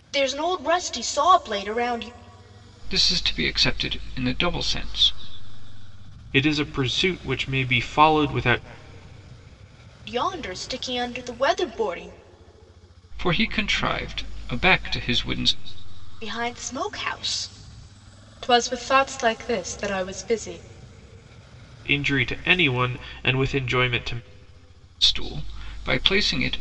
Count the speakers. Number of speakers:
three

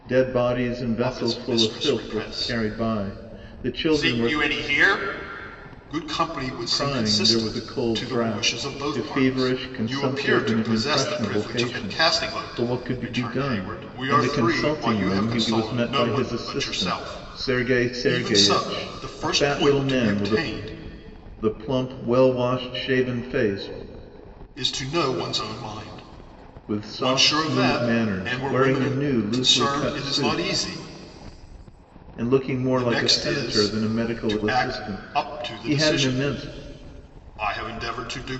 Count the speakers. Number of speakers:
two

